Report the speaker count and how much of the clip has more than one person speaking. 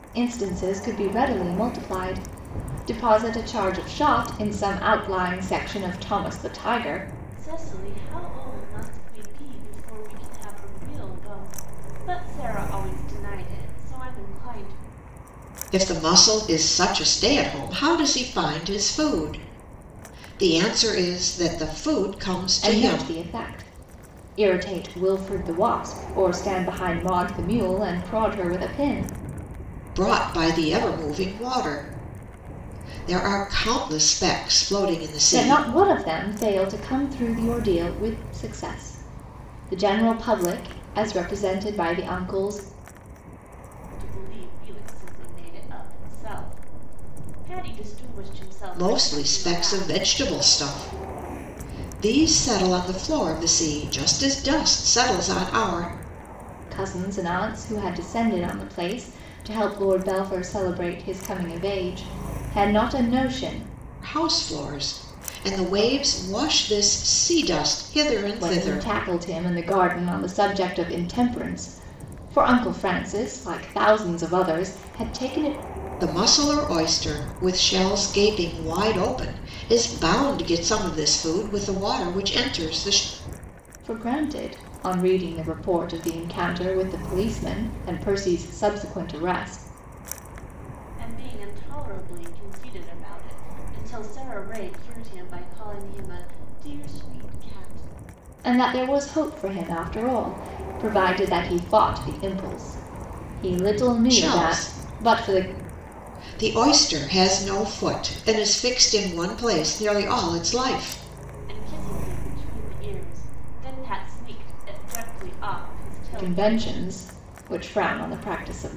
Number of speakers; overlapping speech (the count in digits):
3, about 4%